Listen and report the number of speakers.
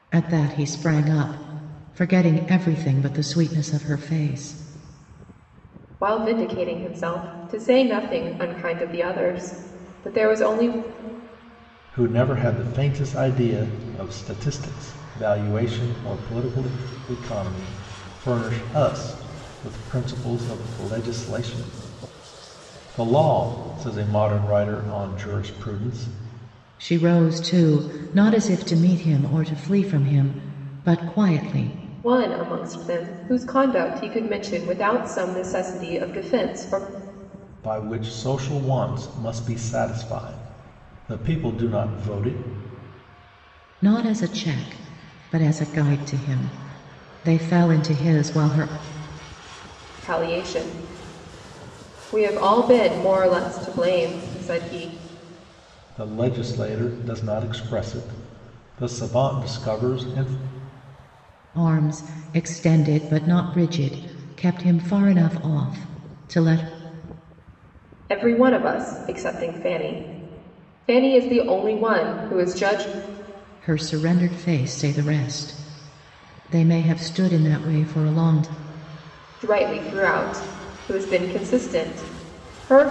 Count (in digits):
3